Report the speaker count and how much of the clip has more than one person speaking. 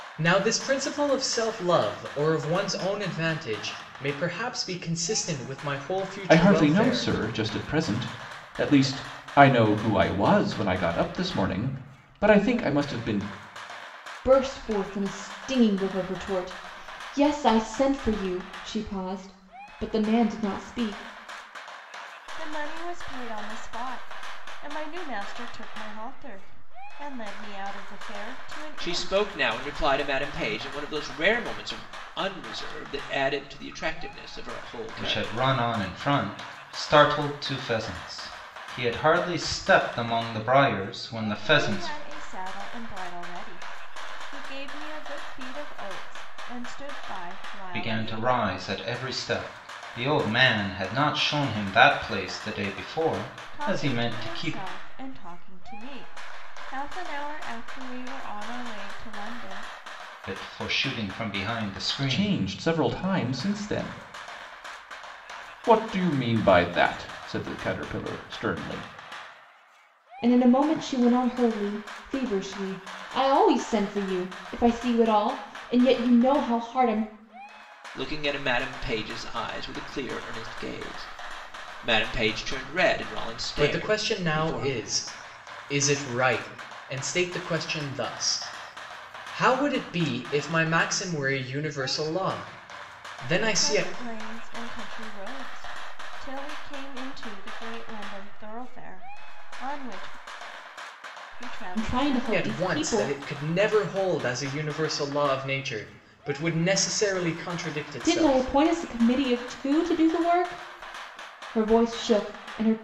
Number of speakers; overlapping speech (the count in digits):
6, about 7%